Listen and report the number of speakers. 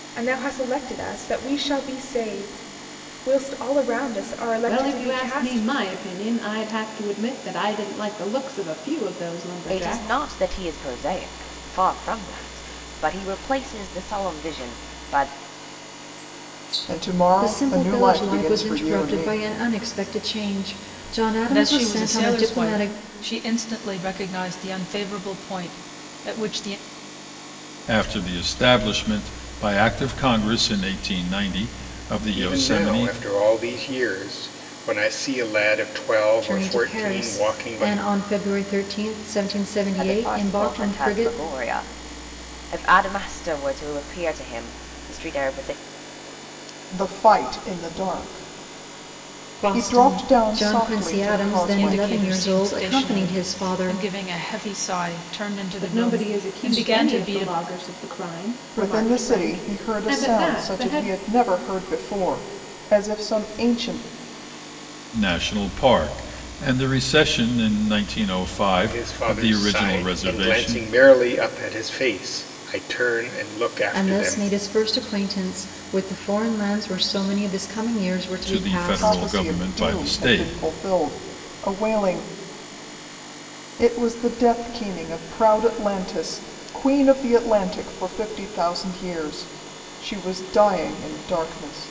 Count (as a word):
eight